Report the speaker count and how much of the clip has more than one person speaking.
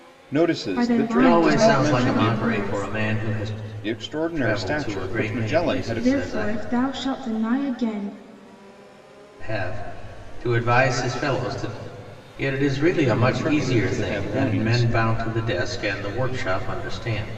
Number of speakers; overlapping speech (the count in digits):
3, about 36%